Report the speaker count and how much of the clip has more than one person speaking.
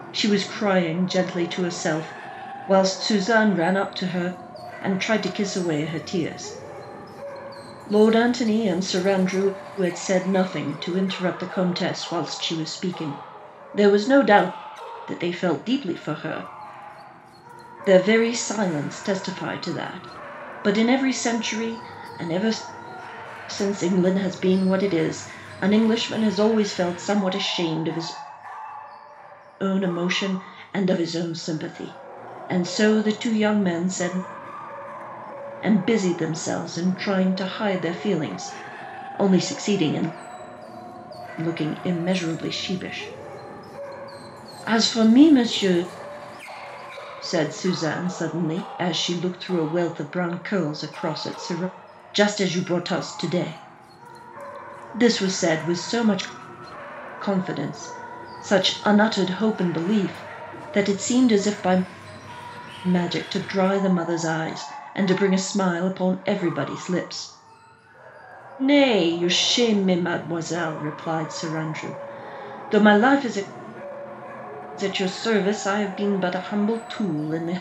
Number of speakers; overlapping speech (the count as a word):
one, no overlap